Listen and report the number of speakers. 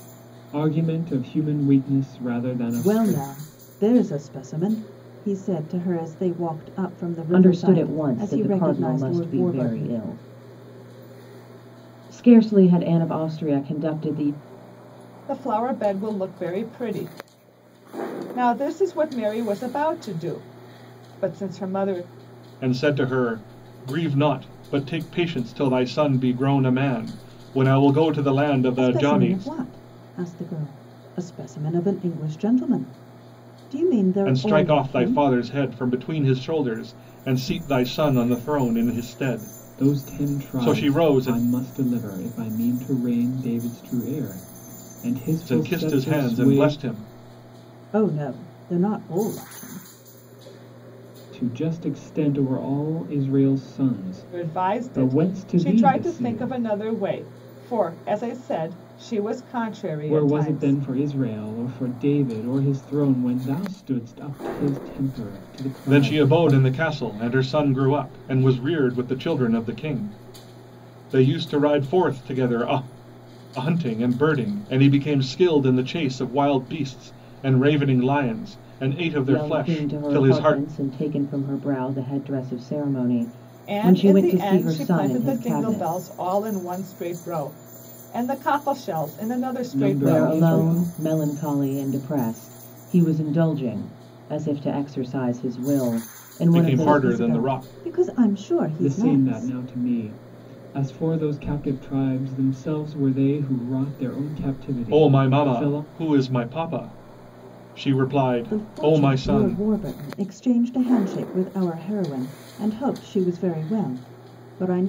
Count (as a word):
five